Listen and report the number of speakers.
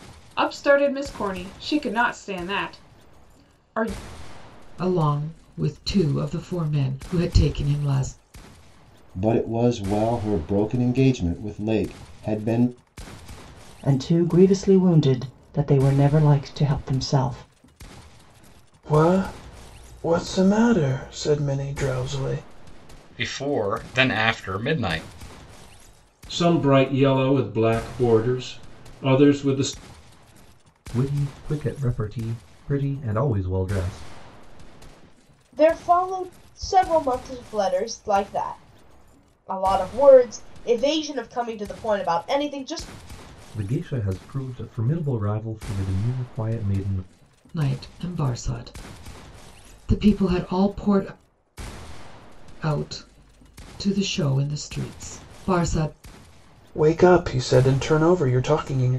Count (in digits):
9